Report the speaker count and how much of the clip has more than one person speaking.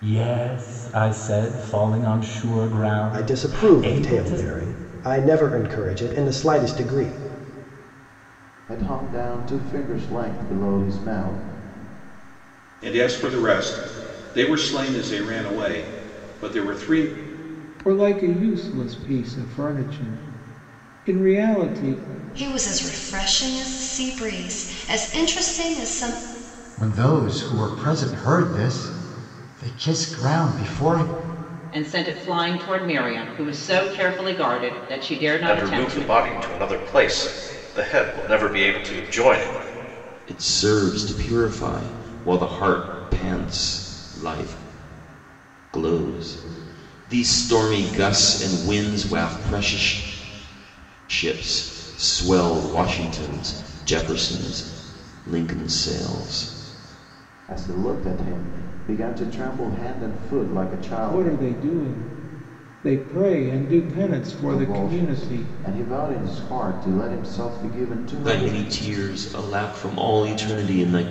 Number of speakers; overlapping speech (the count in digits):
10, about 5%